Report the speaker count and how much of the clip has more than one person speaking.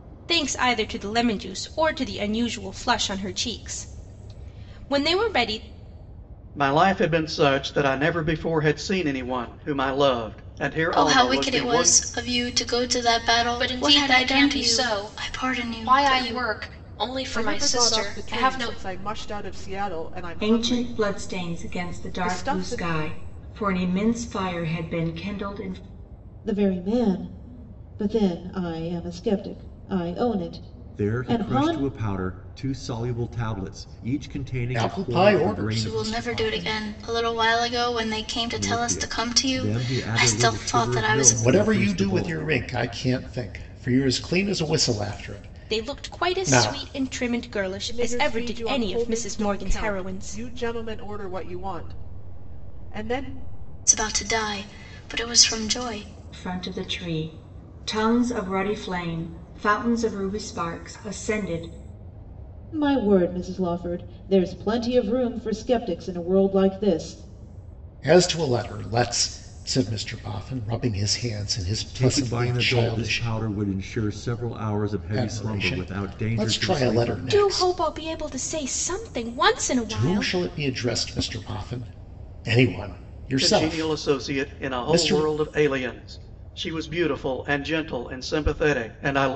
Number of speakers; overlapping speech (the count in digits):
9, about 28%